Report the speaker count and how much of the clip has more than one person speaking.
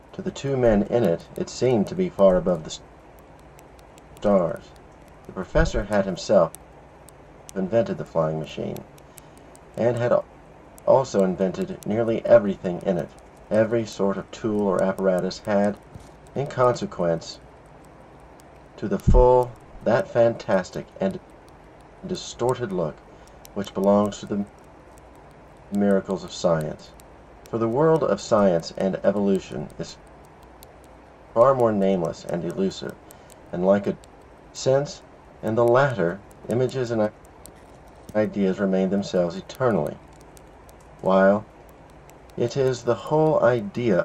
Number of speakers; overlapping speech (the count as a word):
one, no overlap